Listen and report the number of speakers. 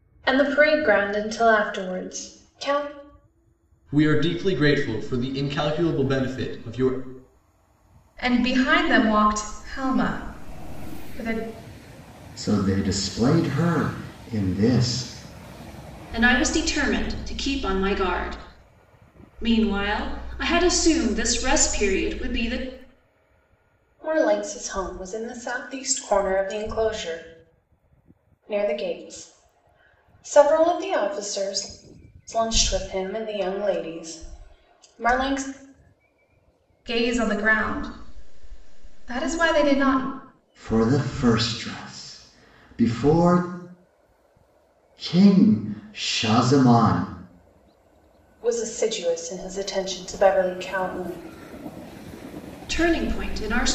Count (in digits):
5